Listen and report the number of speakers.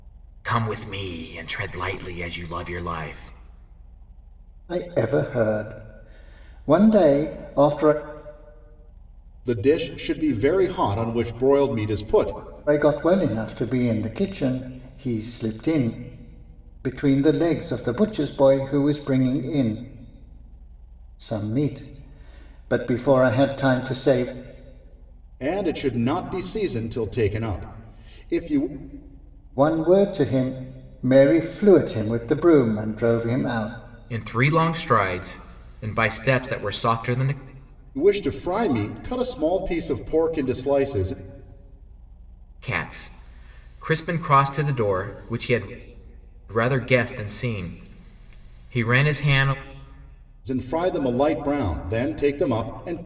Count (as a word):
three